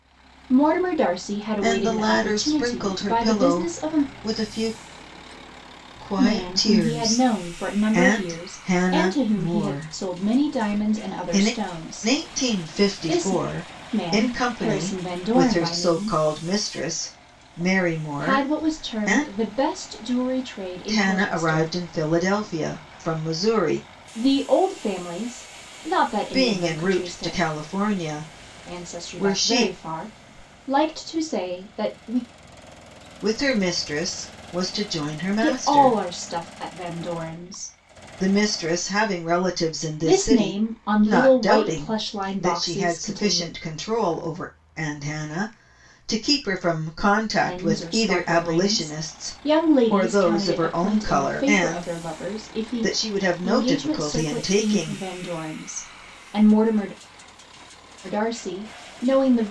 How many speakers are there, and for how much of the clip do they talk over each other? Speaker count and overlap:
2, about 43%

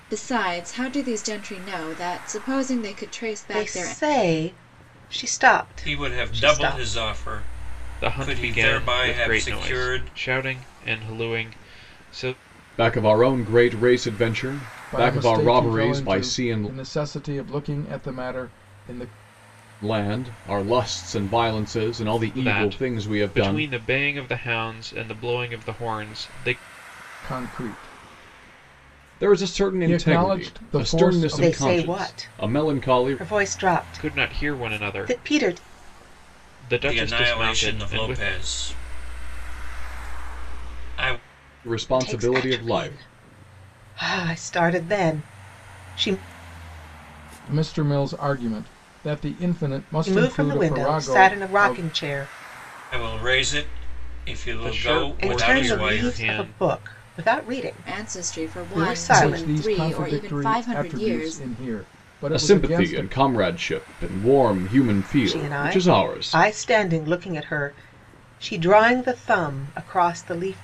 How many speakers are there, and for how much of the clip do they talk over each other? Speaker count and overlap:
6, about 35%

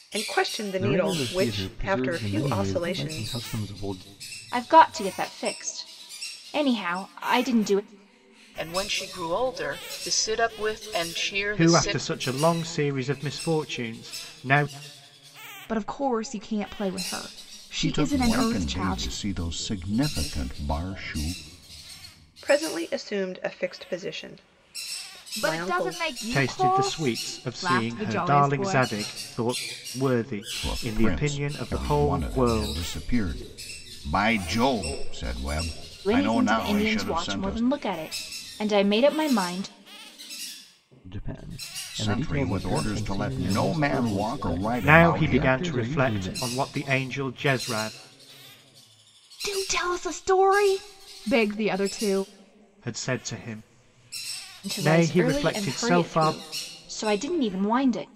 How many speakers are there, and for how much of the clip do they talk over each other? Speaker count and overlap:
7, about 31%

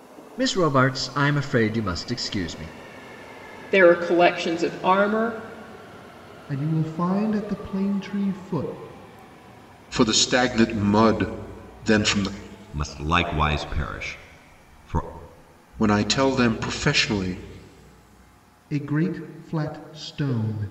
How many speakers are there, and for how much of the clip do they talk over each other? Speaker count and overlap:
5, no overlap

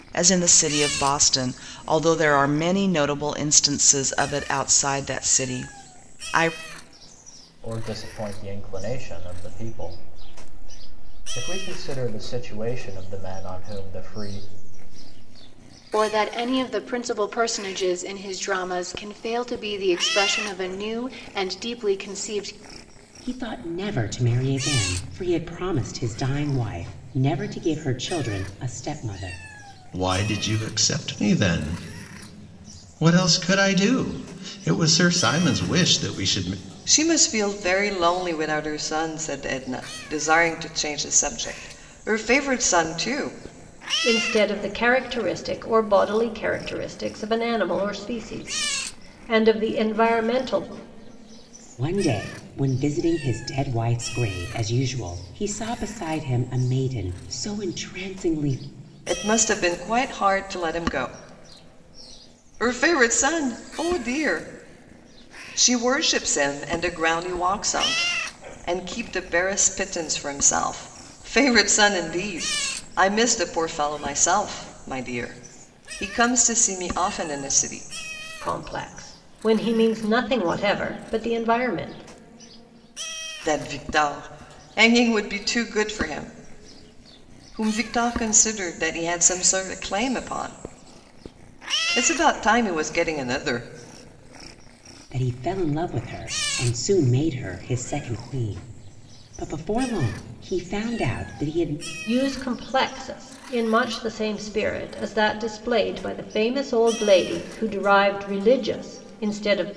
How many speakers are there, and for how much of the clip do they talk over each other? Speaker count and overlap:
7, no overlap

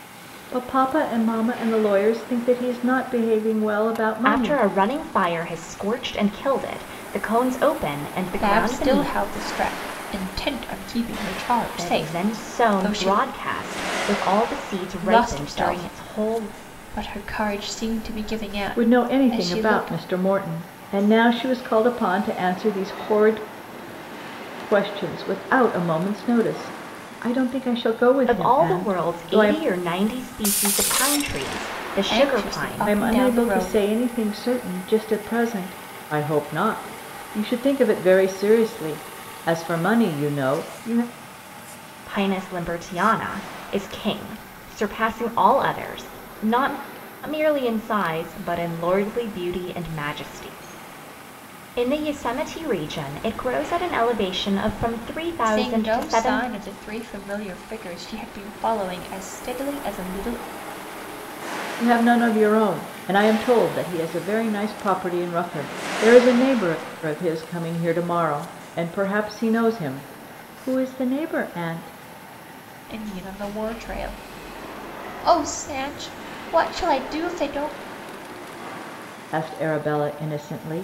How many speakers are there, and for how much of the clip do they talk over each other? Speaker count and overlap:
3, about 12%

